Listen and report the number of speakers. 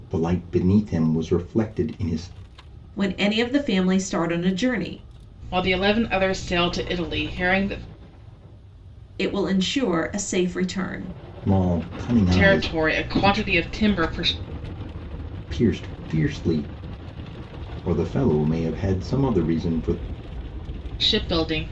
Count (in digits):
3